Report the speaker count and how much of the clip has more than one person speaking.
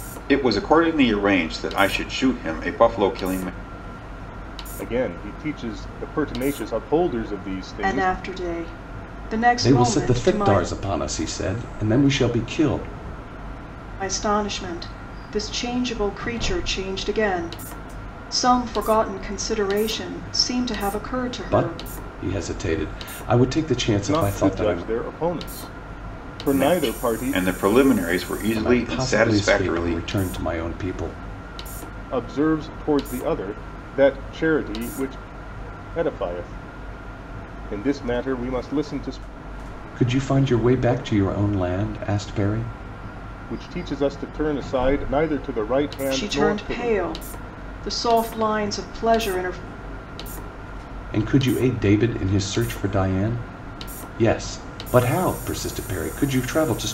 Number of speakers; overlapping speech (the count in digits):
4, about 10%